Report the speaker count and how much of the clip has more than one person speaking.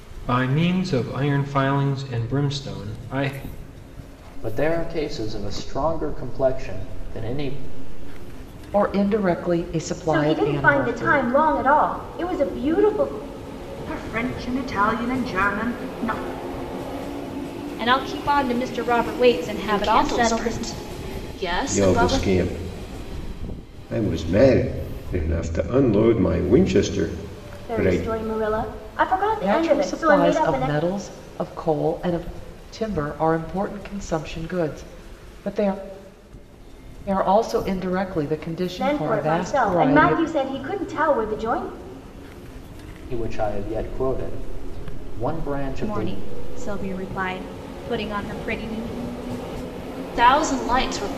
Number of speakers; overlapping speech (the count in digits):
8, about 13%